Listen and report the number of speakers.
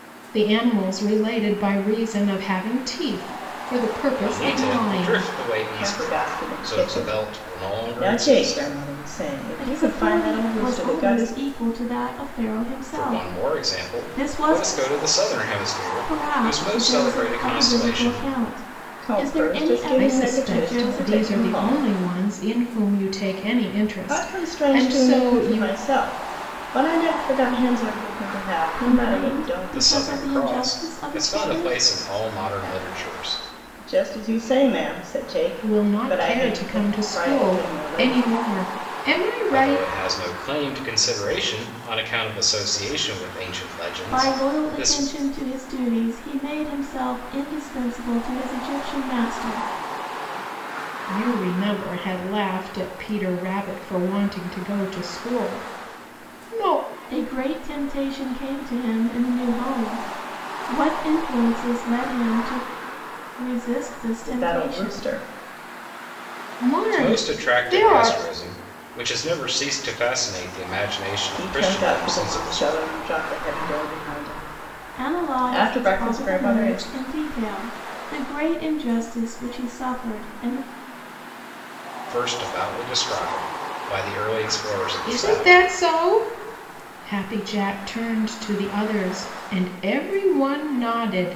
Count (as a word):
four